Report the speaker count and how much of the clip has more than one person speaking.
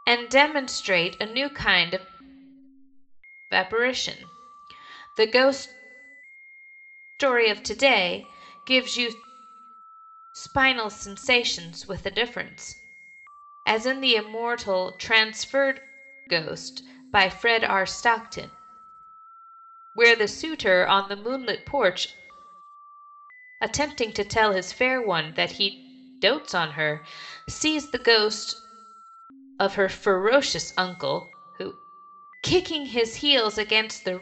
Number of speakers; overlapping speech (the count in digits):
1, no overlap